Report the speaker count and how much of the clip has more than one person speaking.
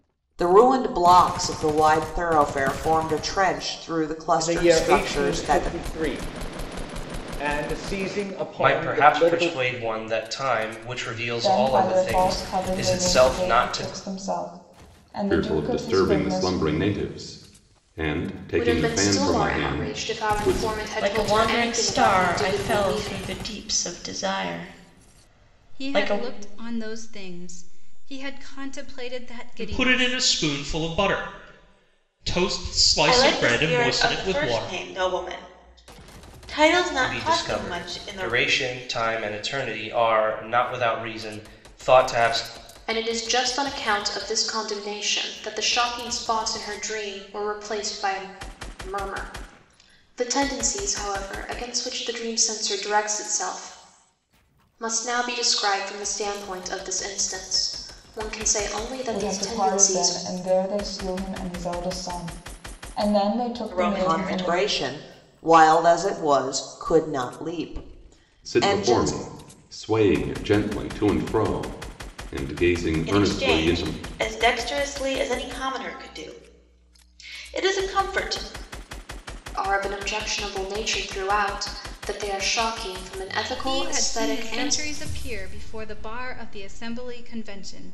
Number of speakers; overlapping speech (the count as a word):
ten, about 23%